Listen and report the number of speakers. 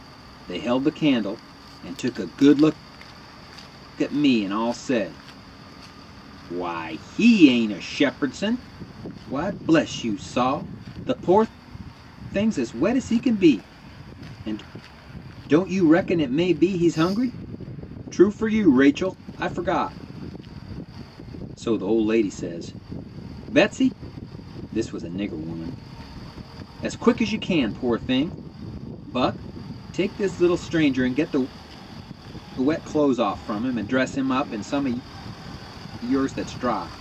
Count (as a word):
one